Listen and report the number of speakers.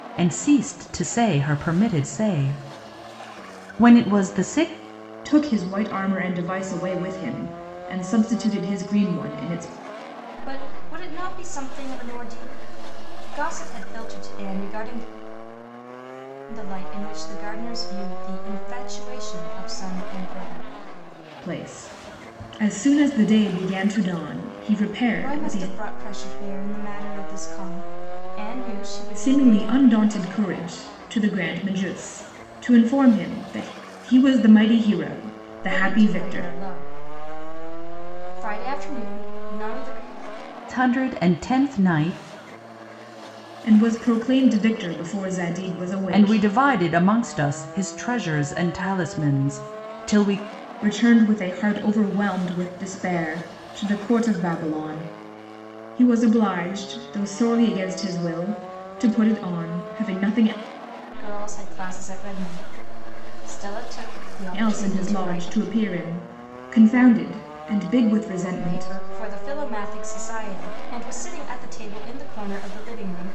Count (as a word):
three